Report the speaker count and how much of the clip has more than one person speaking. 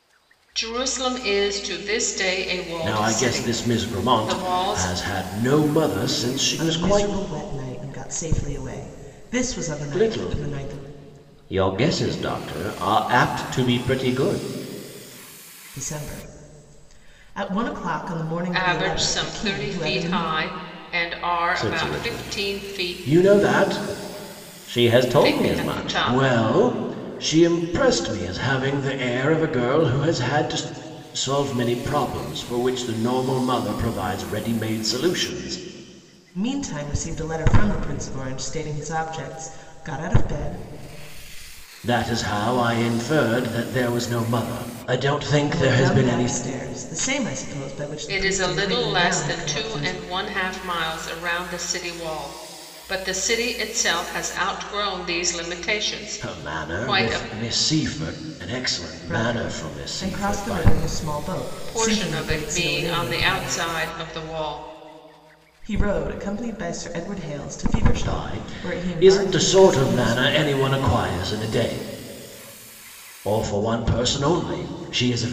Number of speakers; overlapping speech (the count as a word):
three, about 24%